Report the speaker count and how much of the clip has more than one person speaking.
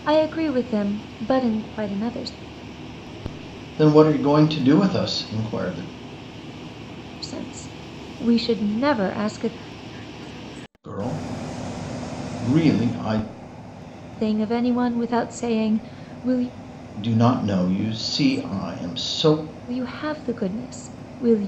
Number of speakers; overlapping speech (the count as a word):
two, no overlap